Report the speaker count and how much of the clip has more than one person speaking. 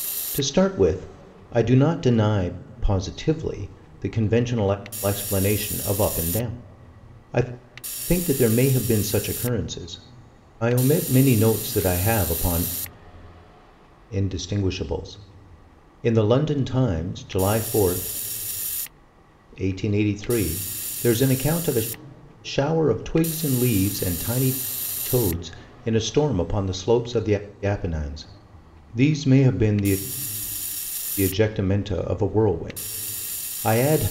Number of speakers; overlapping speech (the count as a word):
one, no overlap